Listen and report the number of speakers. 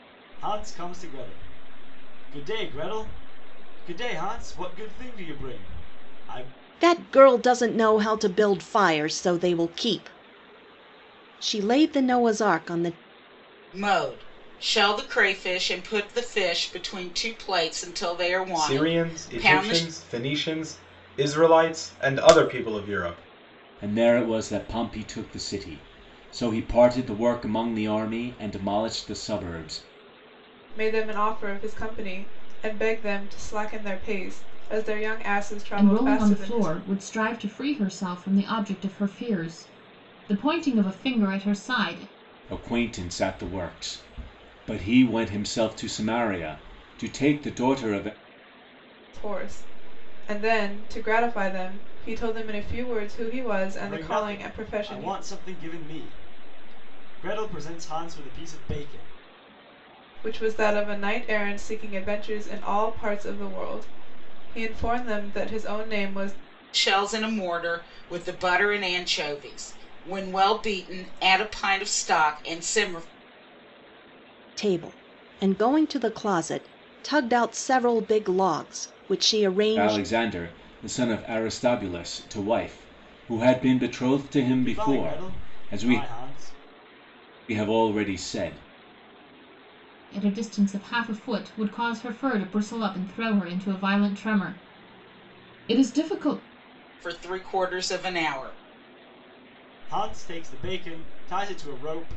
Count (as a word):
seven